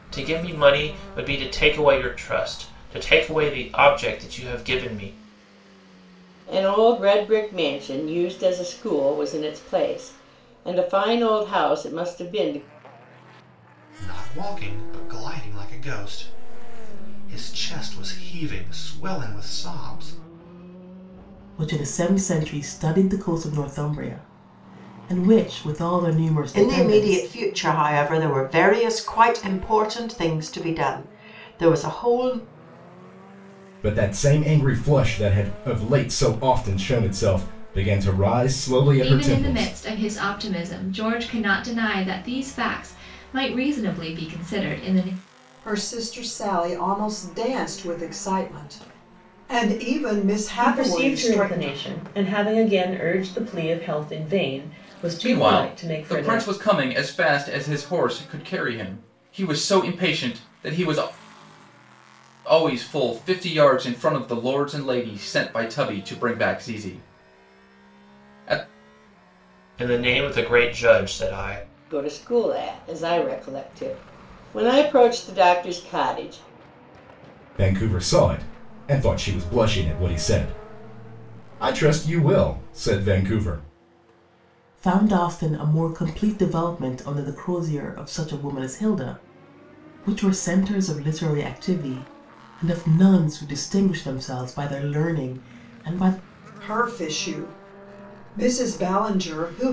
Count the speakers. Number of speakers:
ten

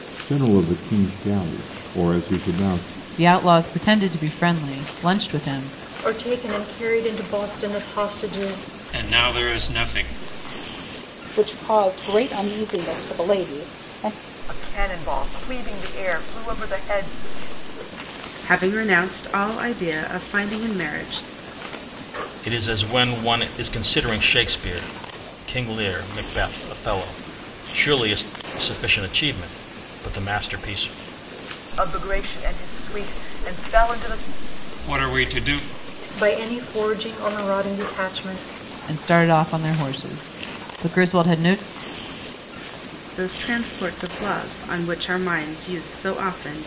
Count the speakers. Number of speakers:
eight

